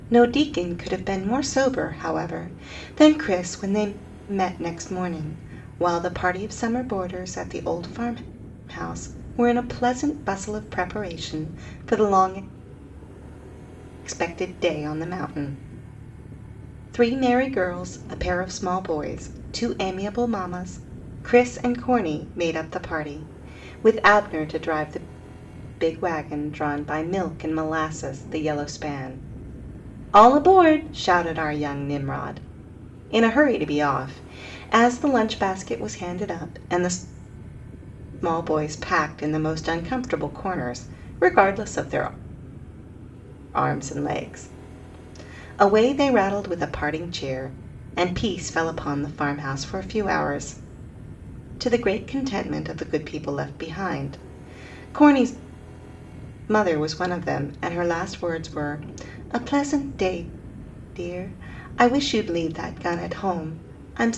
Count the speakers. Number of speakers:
1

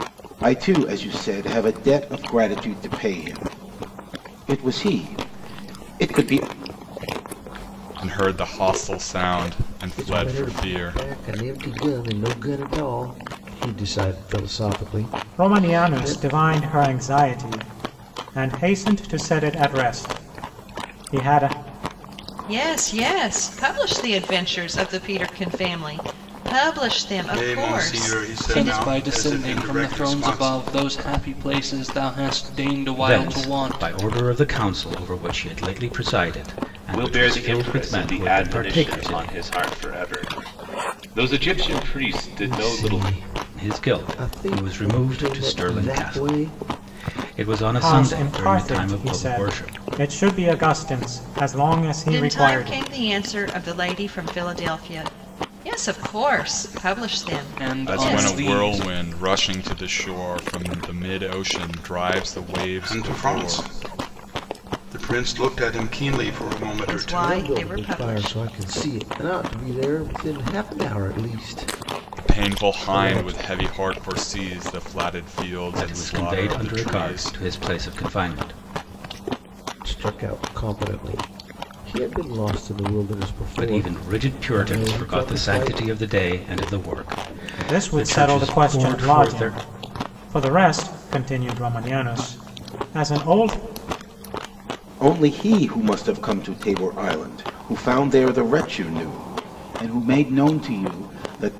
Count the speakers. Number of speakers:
9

